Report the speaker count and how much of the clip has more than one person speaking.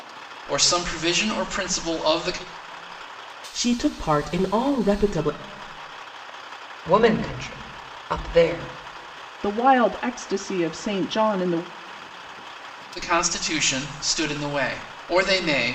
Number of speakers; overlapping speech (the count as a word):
four, no overlap